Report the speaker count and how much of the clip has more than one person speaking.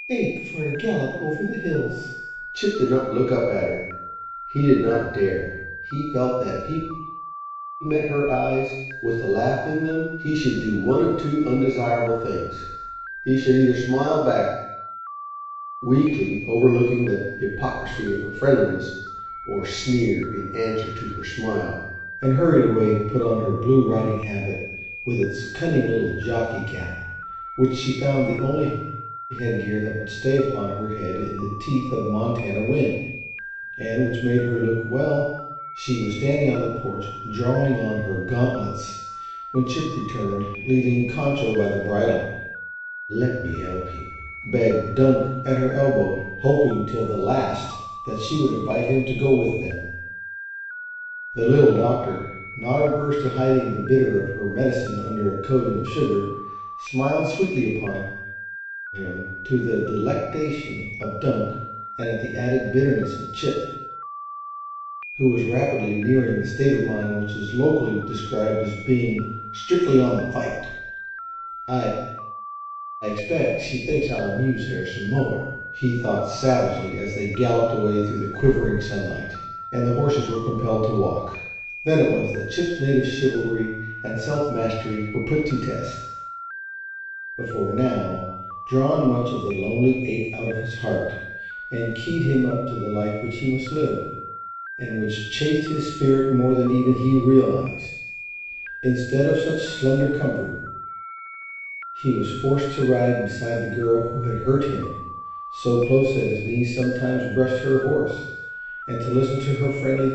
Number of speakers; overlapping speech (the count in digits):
1, no overlap